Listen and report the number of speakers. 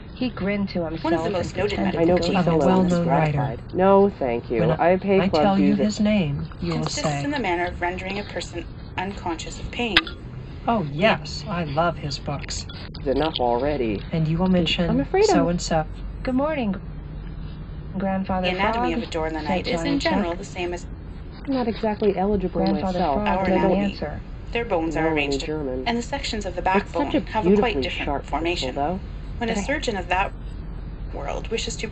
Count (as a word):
four